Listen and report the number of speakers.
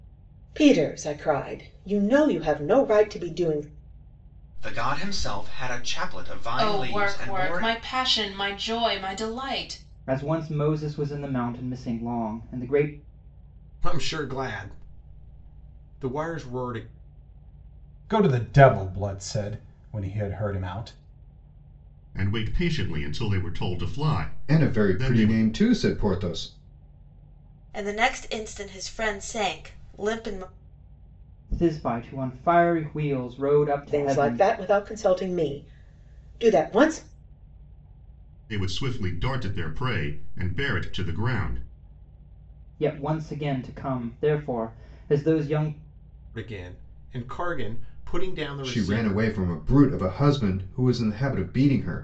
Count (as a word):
nine